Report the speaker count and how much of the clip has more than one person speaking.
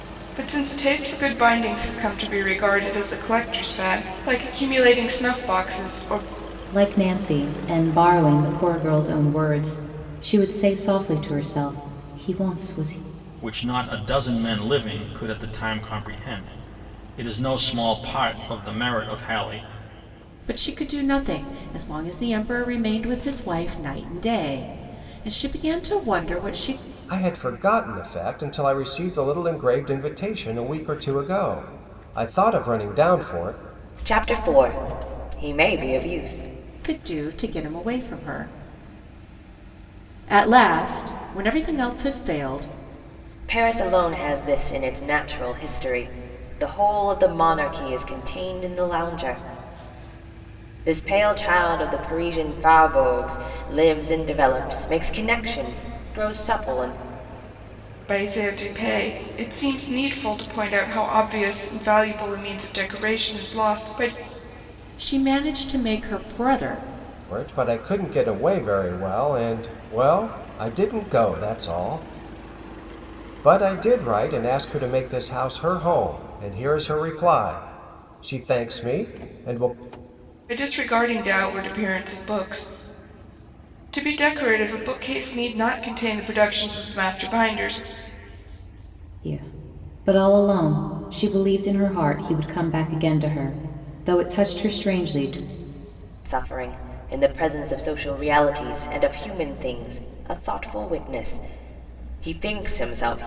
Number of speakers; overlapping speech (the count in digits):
6, no overlap